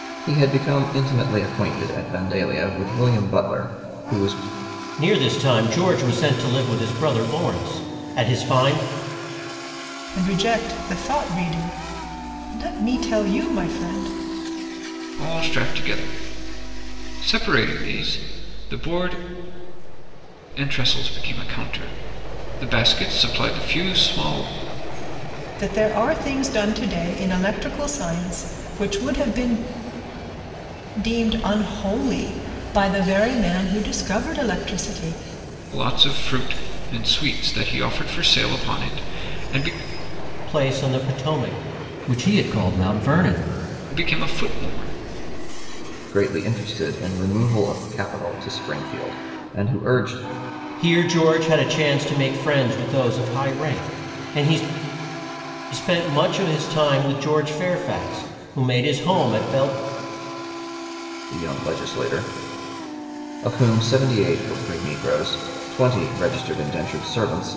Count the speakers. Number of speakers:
four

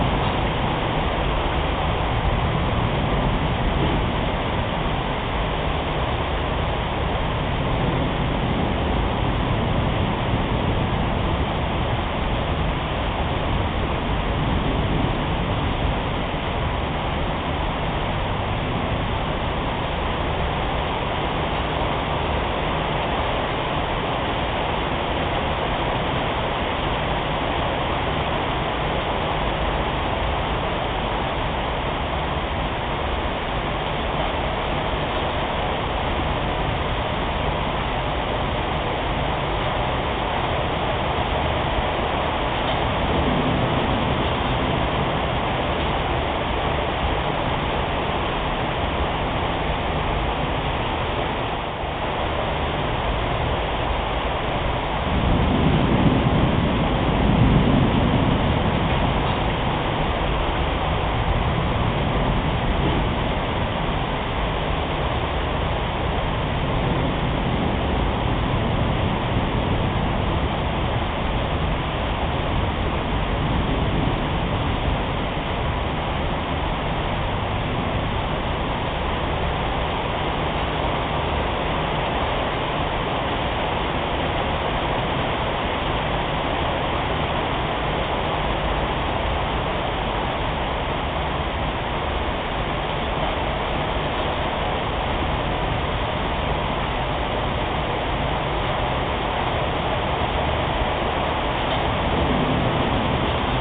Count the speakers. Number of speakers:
zero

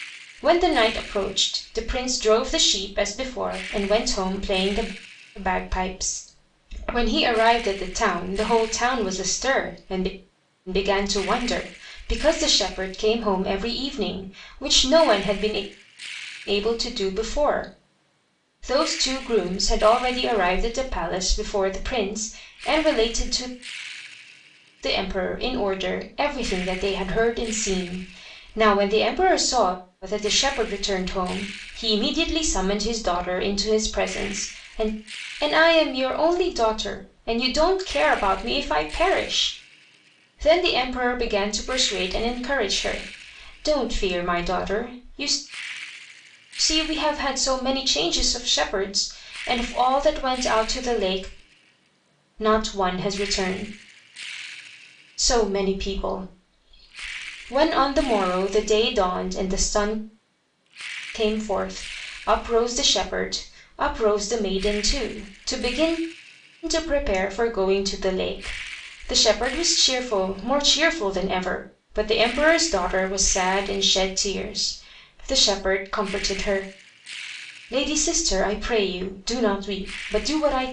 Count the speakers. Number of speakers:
one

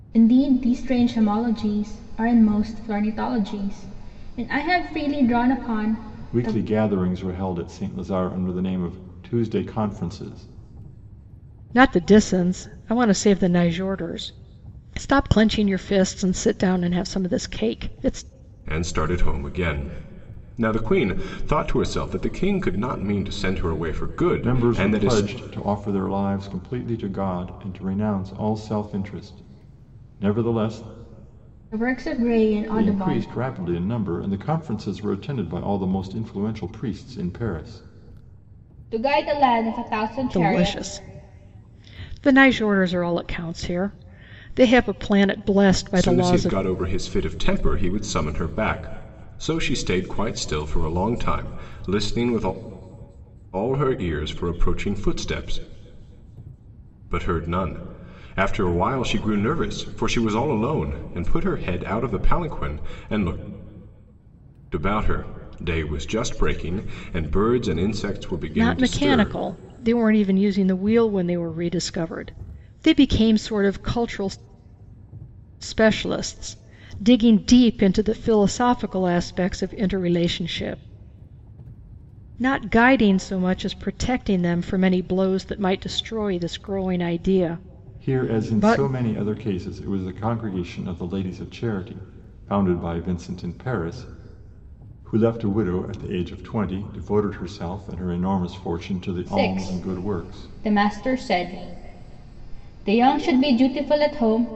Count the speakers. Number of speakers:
four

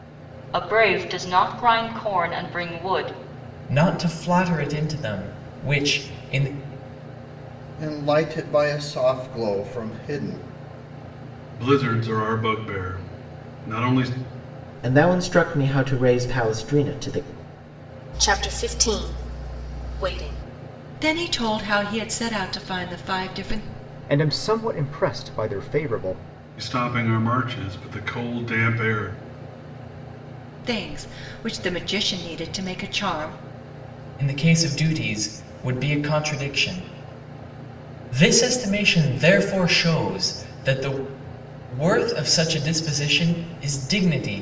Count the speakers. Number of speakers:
eight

